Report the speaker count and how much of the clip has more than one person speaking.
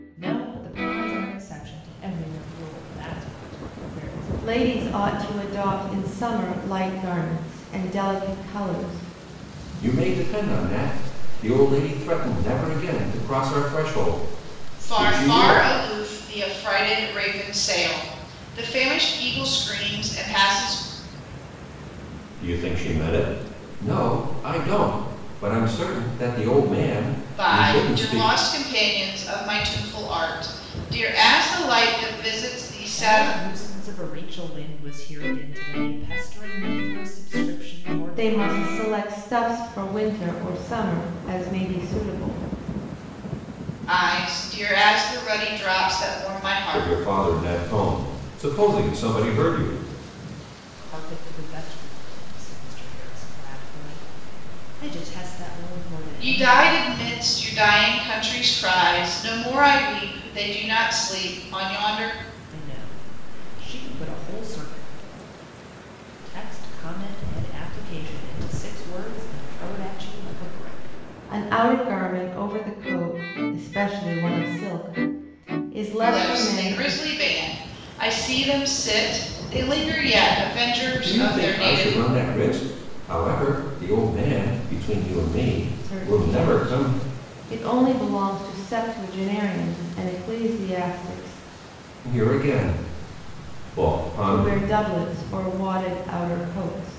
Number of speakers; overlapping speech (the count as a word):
four, about 9%